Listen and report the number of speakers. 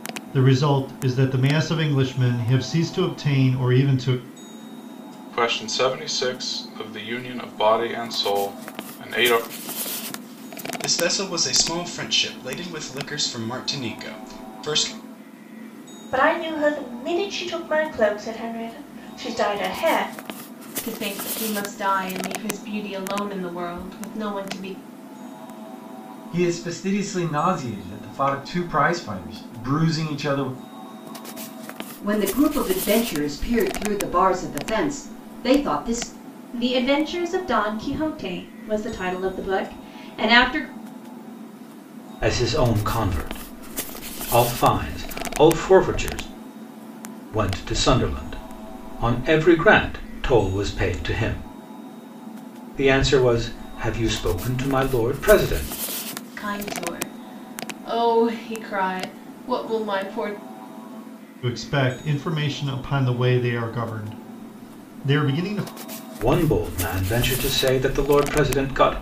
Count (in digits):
9